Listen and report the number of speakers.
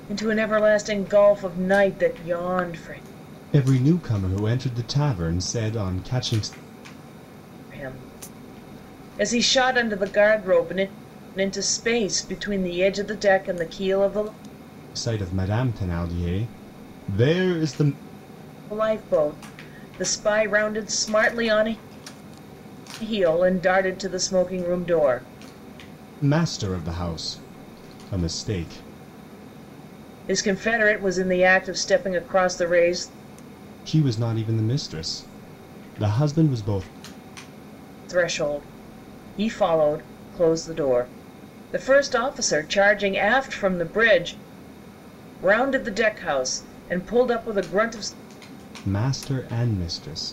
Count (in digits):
2